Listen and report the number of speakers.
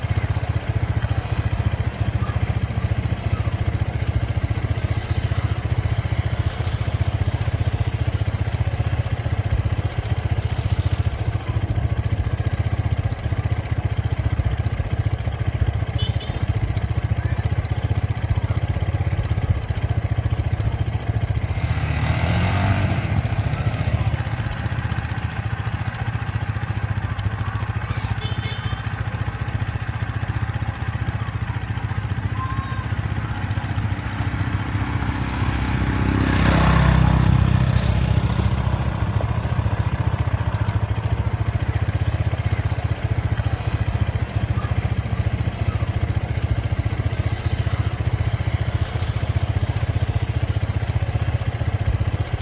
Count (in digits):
0